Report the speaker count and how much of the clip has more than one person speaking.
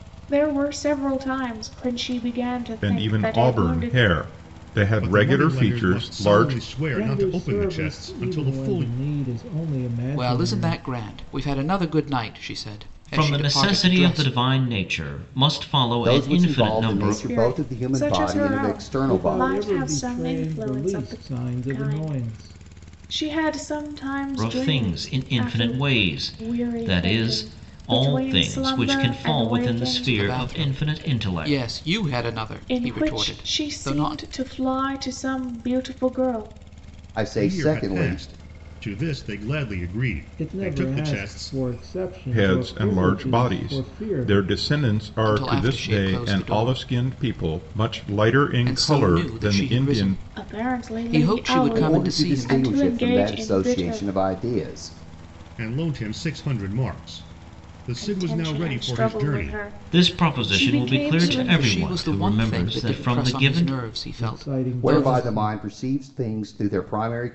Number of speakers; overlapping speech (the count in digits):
7, about 58%